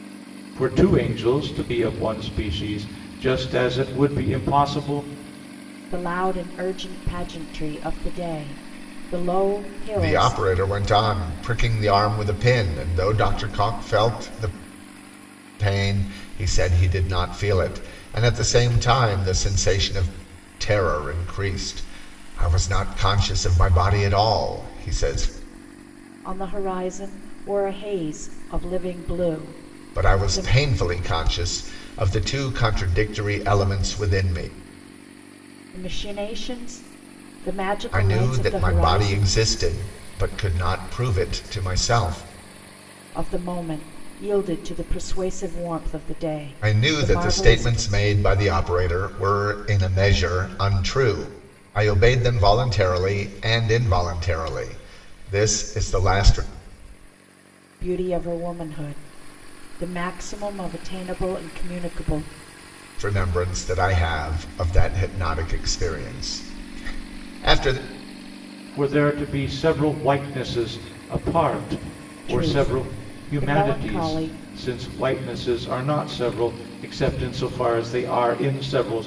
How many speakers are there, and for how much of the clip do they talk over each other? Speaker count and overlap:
3, about 7%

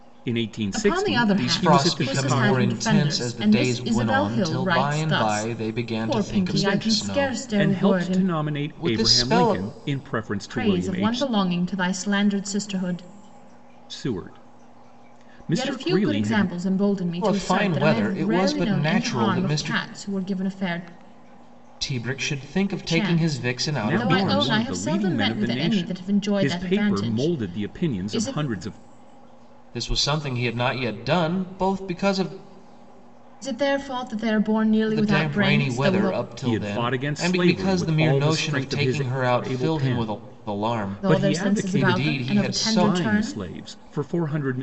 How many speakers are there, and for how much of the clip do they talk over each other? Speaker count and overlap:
3, about 58%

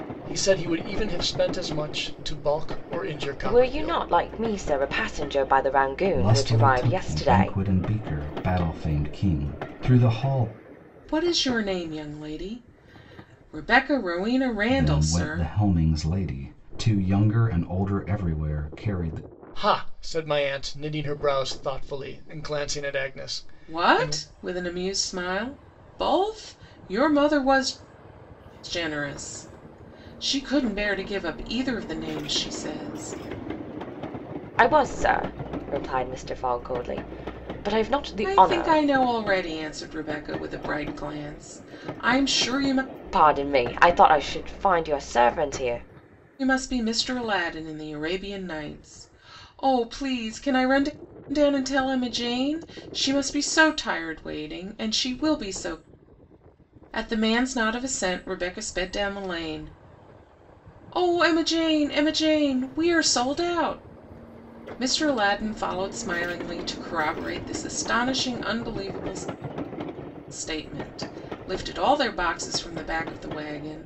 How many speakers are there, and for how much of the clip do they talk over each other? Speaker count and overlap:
4, about 5%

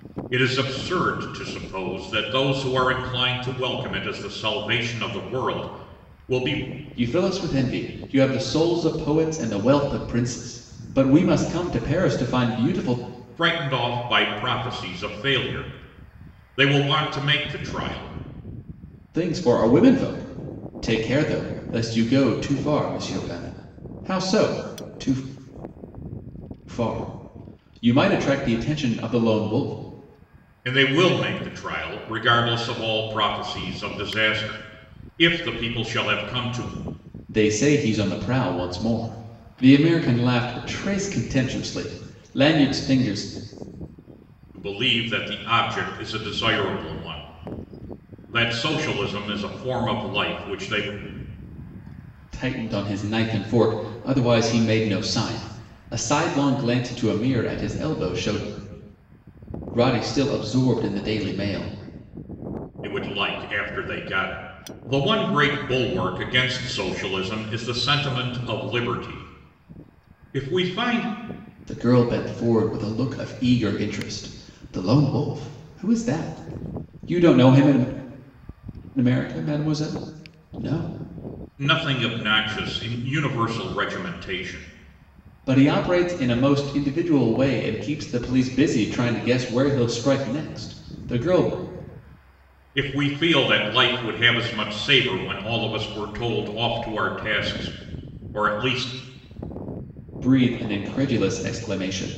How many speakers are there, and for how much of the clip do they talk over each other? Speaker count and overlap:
2, no overlap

